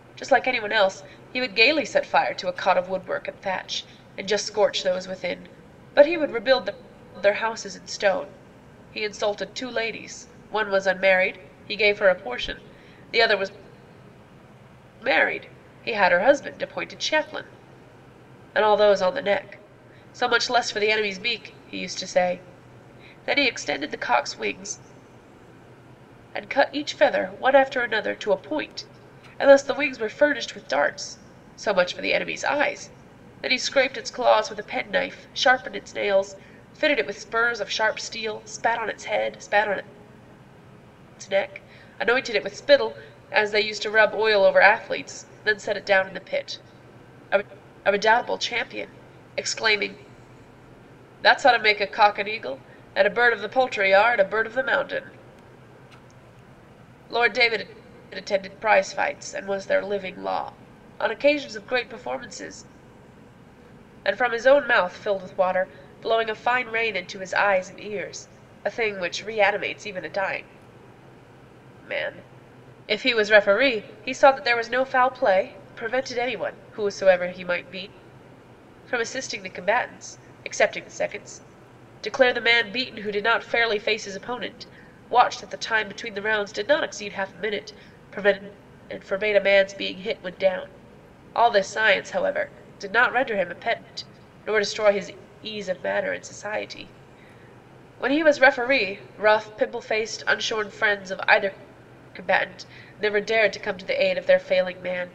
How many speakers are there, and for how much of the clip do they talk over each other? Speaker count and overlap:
one, no overlap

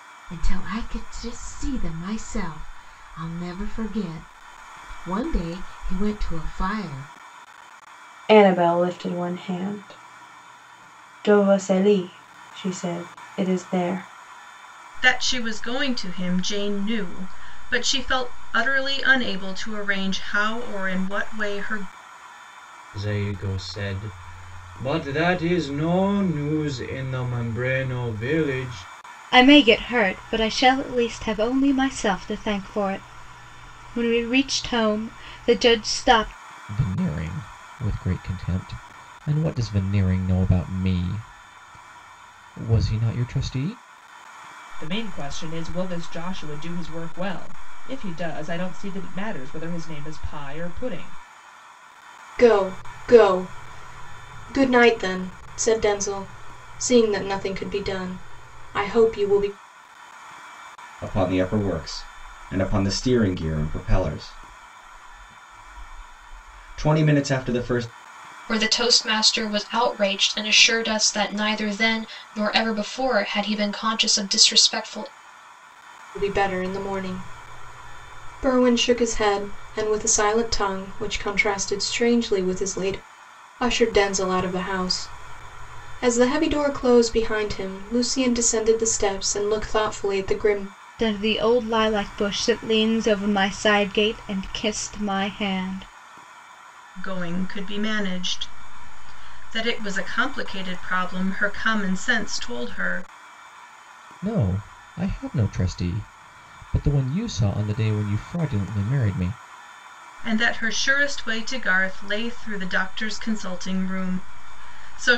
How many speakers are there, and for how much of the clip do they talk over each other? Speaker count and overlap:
ten, no overlap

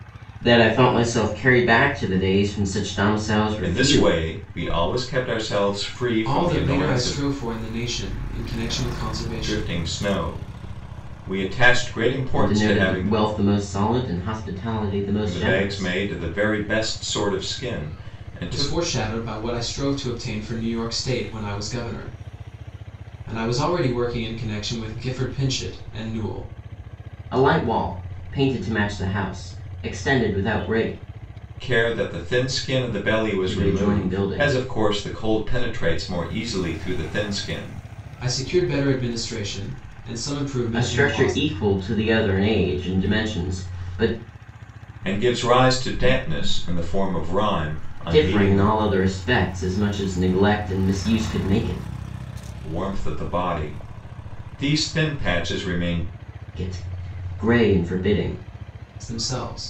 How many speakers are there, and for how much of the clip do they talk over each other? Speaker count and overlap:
three, about 10%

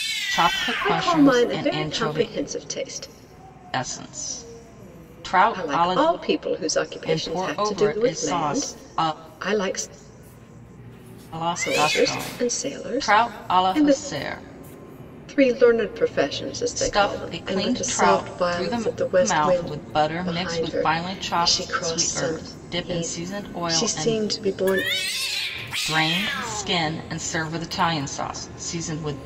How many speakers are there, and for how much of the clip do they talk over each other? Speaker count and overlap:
two, about 43%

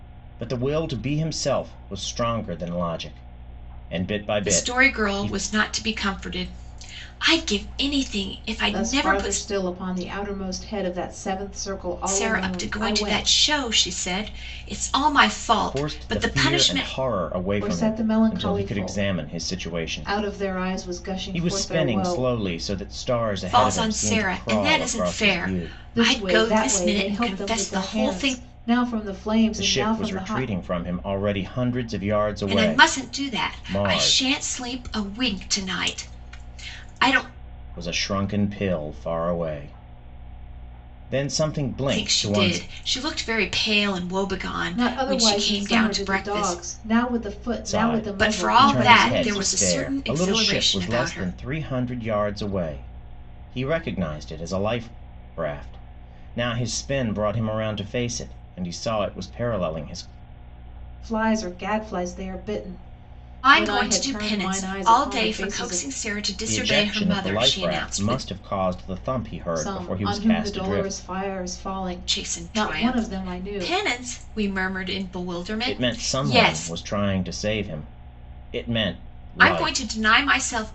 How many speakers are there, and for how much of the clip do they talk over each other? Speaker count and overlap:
three, about 39%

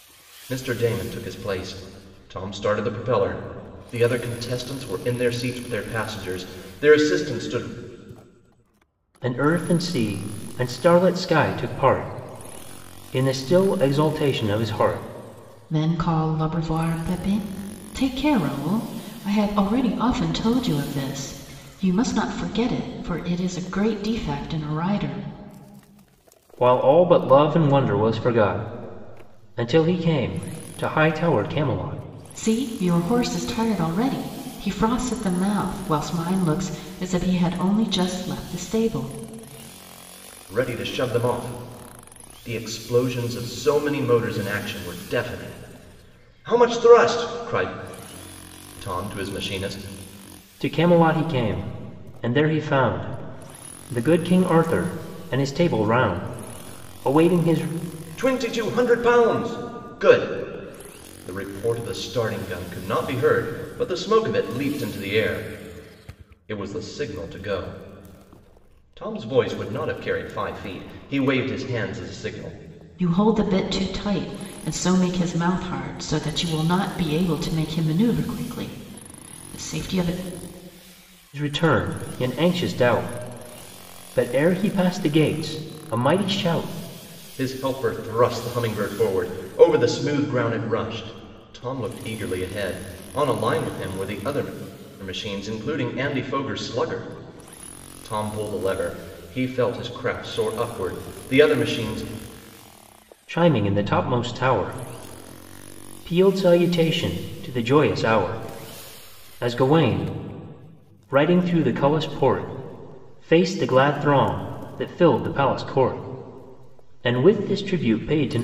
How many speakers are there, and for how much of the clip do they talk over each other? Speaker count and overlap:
three, no overlap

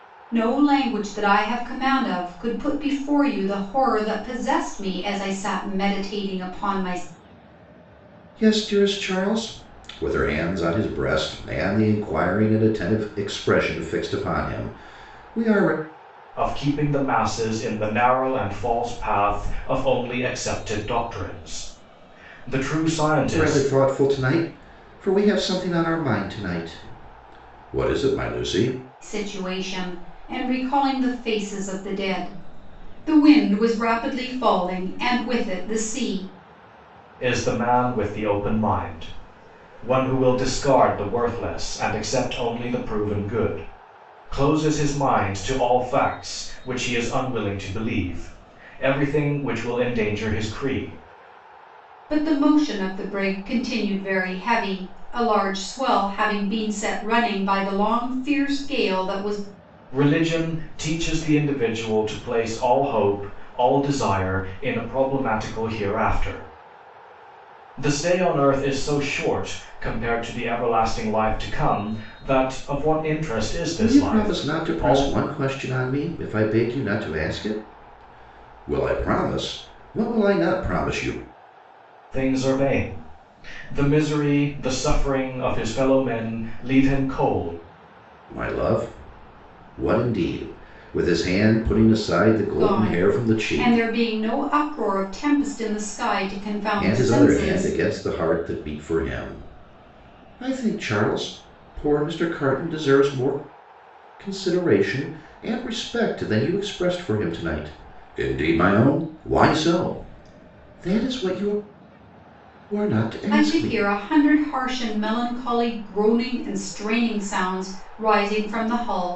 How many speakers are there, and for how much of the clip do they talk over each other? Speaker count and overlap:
three, about 4%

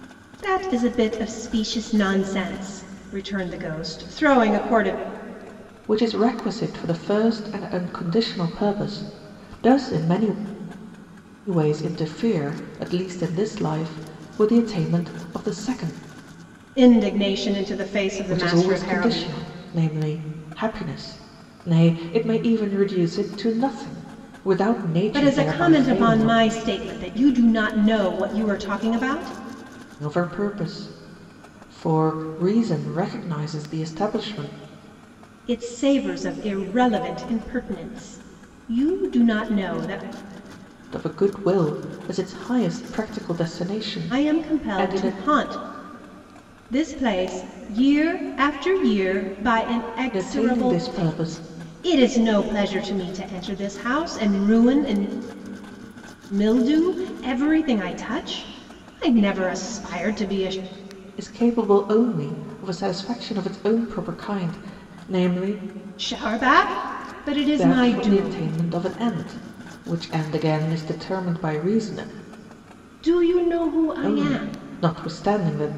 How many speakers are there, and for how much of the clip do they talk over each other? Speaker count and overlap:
two, about 8%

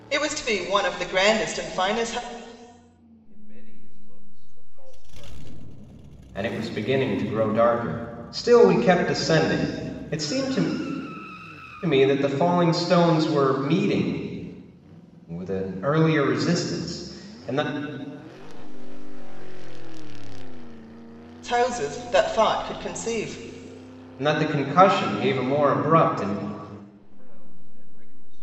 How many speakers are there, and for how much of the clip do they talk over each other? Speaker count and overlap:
three, no overlap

